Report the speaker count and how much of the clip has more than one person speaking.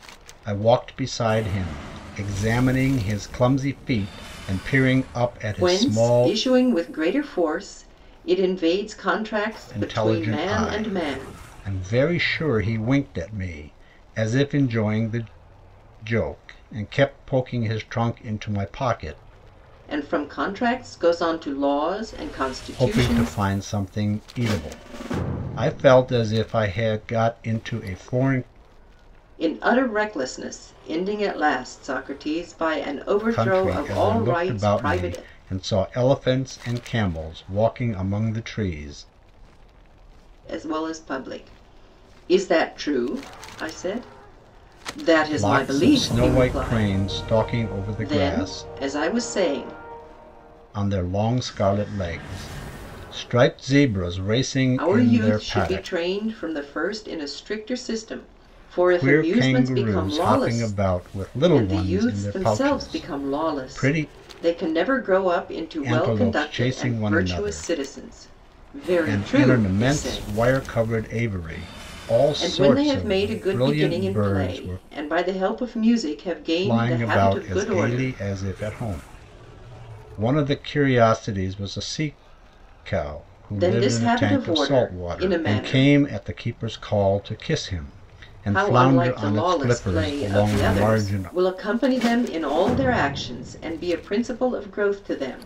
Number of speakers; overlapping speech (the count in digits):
2, about 28%